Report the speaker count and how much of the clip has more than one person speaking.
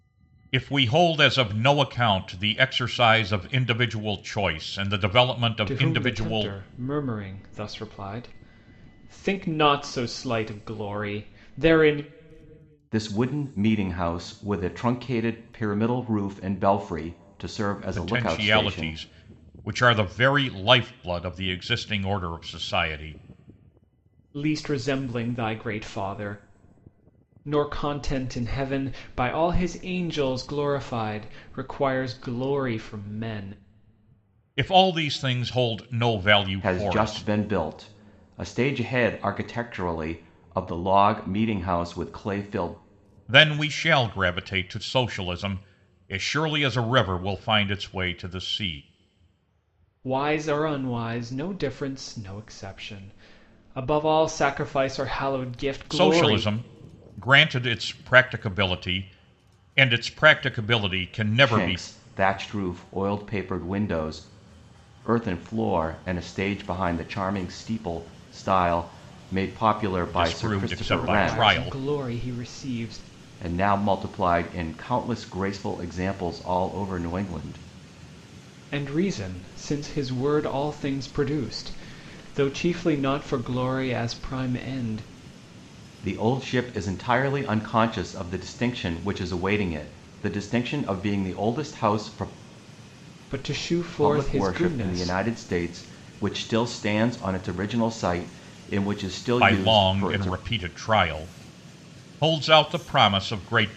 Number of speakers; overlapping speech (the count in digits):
3, about 7%